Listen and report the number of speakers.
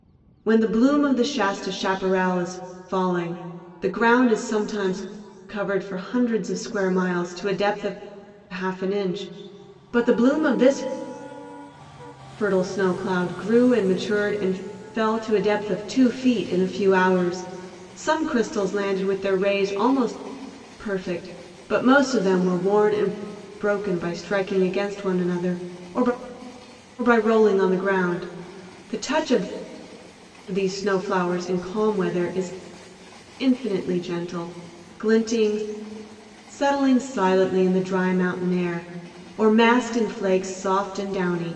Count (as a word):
one